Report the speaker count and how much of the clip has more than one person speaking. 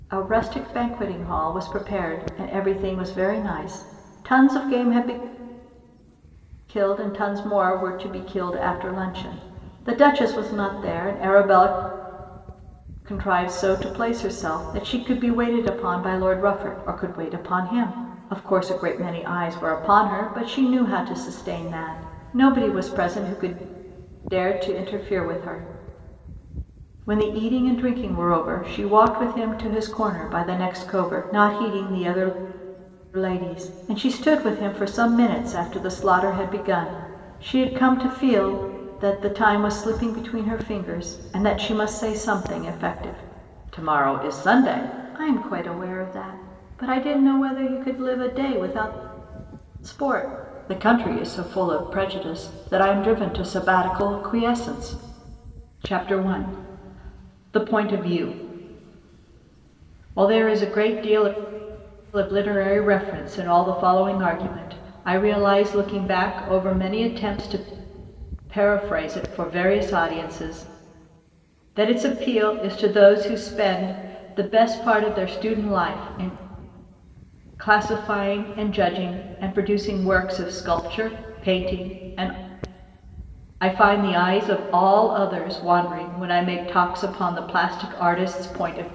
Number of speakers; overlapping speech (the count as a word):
one, no overlap